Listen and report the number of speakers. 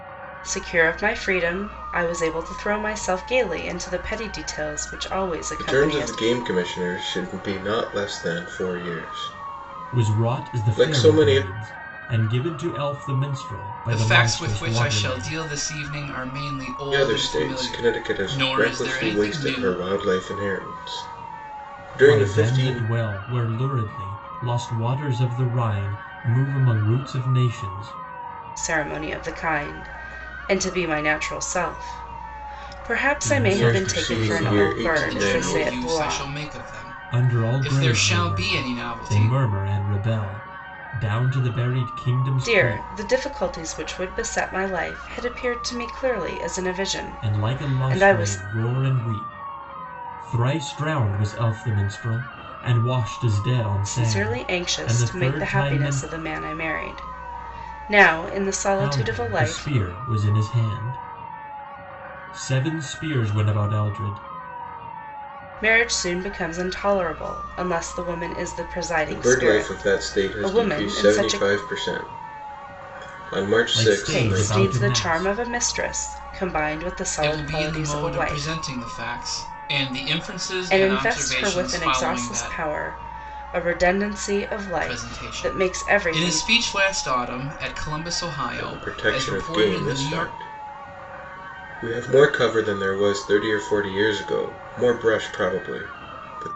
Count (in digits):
4